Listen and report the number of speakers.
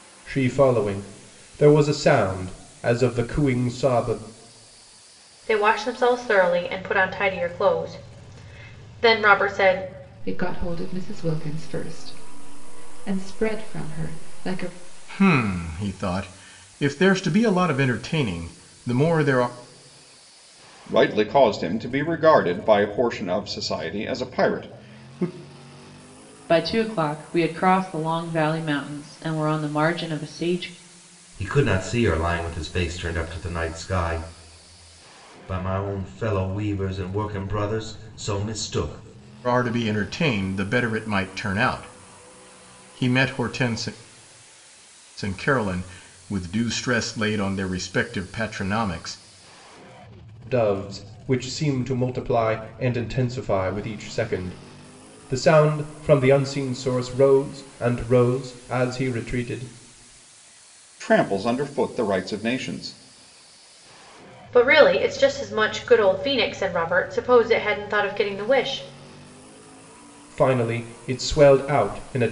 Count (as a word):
seven